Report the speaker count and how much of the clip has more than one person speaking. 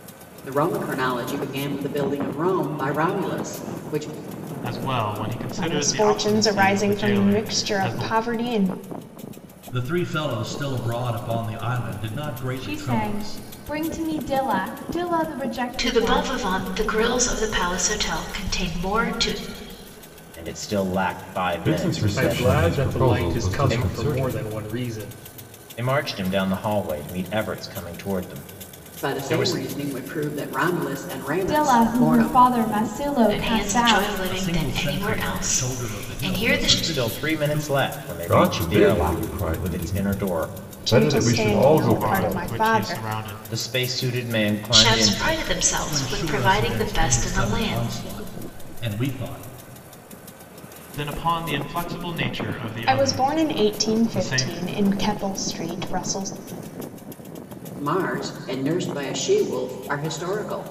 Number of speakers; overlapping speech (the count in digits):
9, about 37%